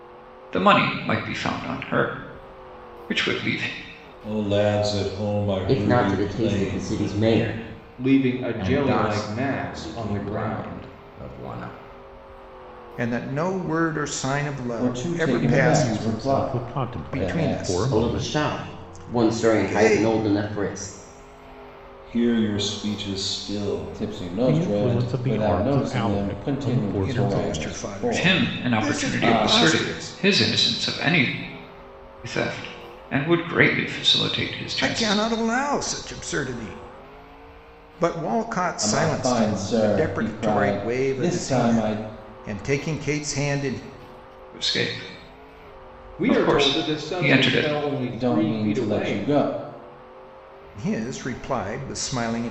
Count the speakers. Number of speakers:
8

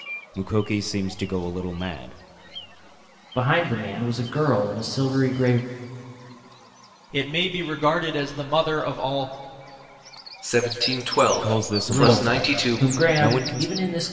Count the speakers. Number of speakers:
4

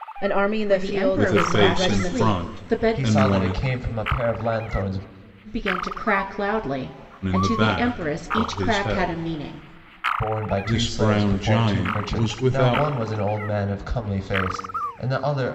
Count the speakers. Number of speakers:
4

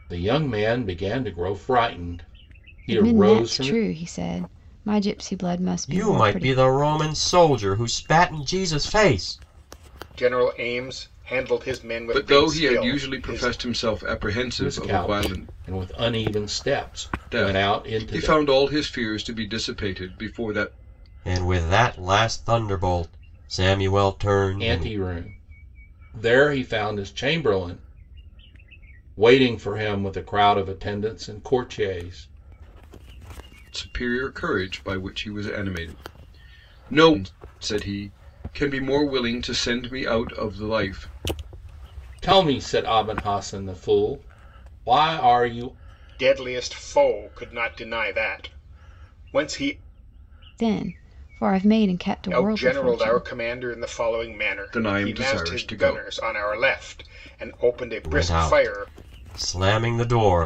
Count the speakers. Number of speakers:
5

